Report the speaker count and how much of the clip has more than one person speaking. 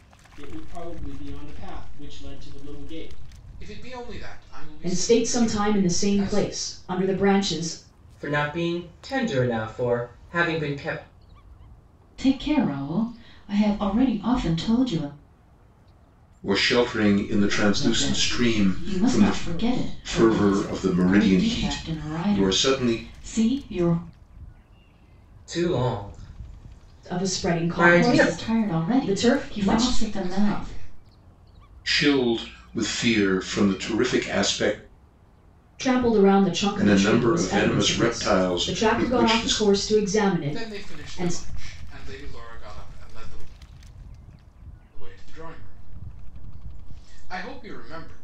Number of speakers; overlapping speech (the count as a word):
six, about 30%